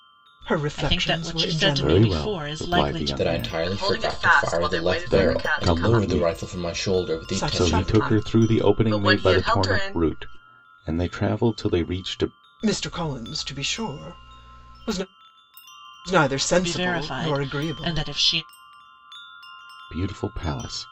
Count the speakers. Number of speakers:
five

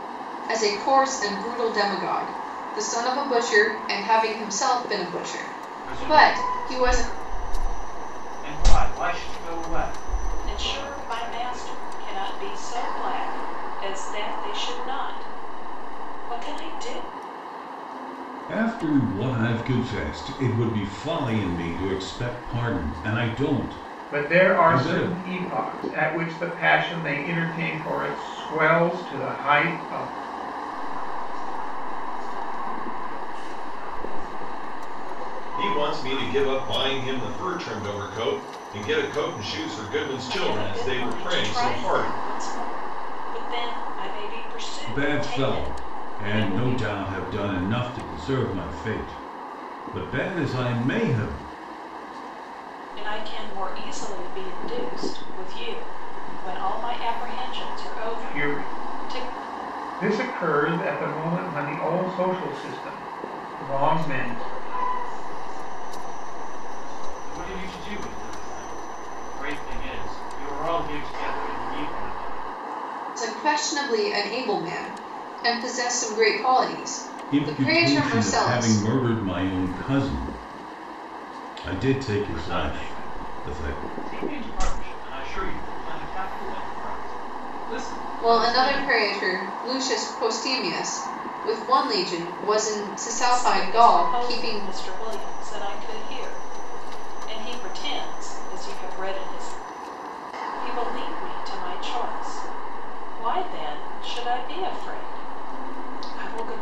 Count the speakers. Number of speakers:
seven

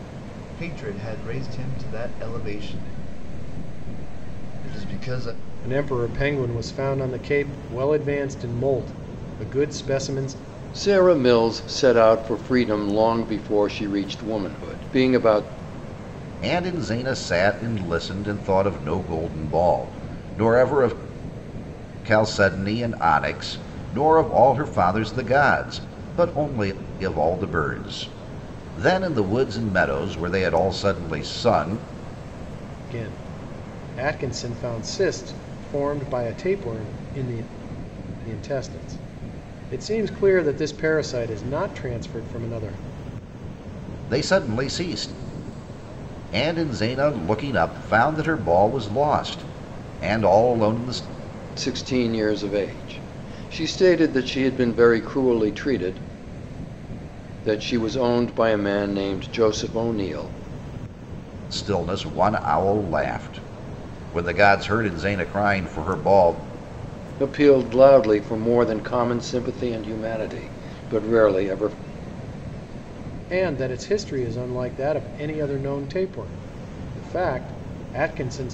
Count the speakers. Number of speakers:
four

